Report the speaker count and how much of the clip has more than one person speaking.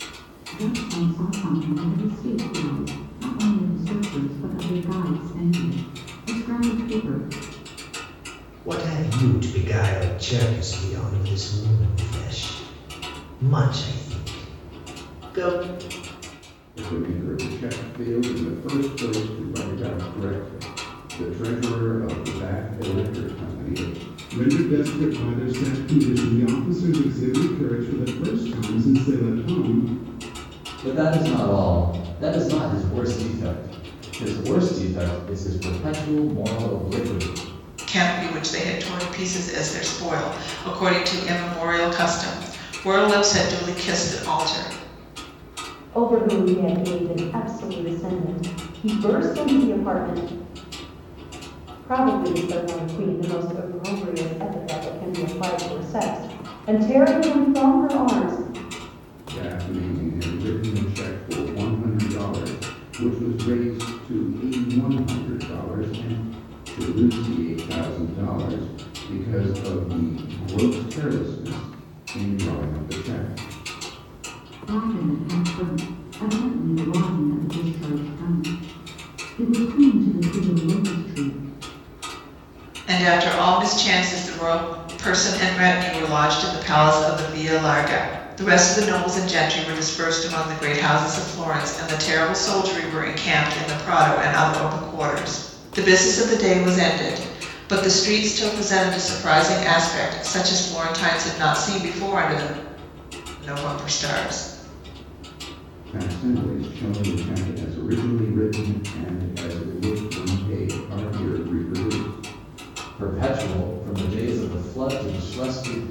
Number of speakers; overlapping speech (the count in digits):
7, no overlap